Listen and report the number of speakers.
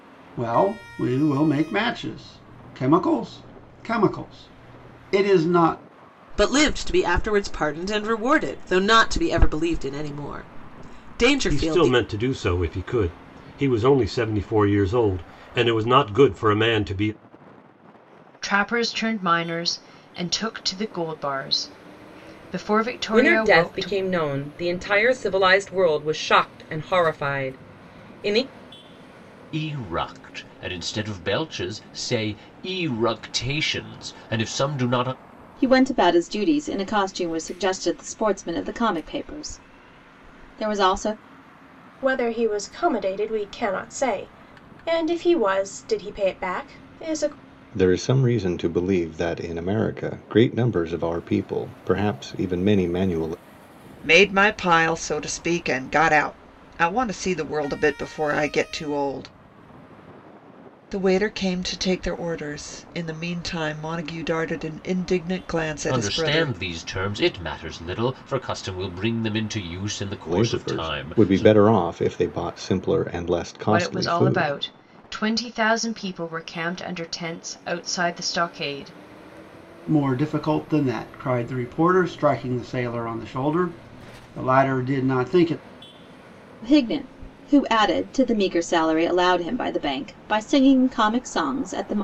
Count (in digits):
10